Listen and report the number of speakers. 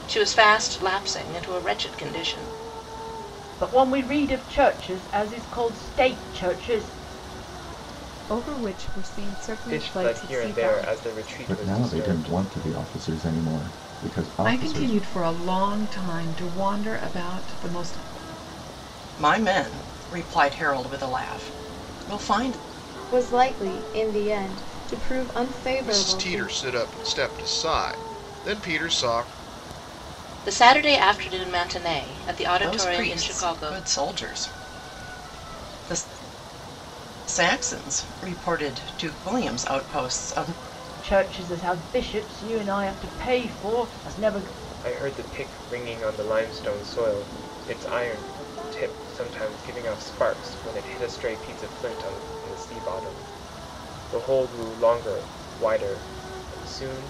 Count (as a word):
nine